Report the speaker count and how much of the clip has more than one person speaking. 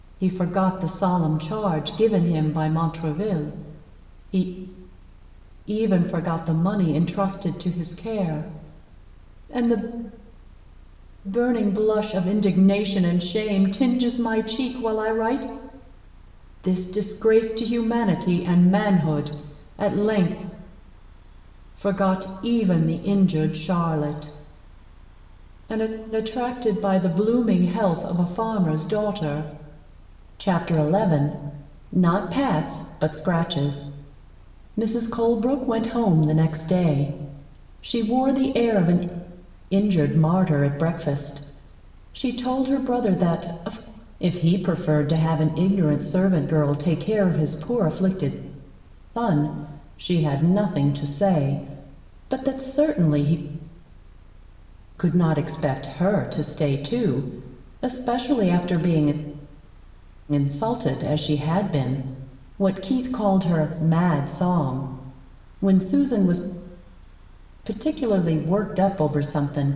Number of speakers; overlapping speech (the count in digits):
1, no overlap